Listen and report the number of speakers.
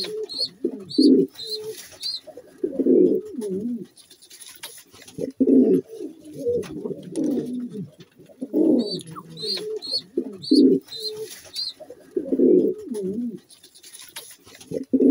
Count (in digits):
0